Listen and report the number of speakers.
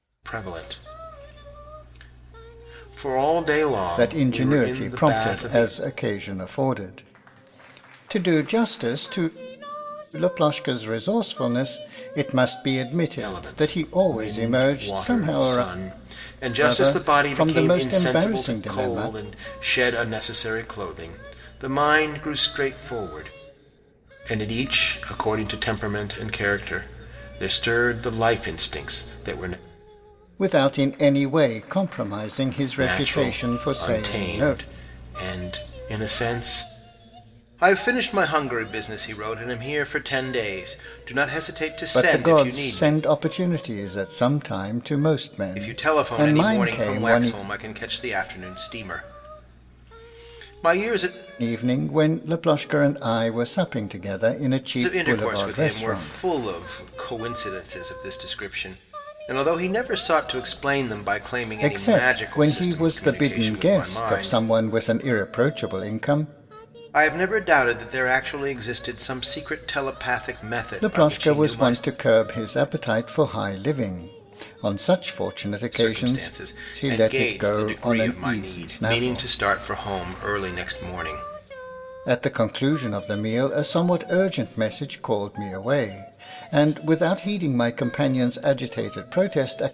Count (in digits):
2